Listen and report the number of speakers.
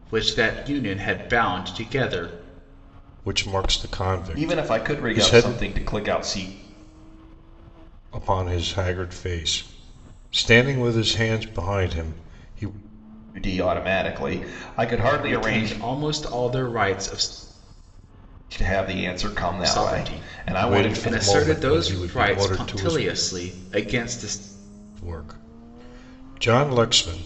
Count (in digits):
3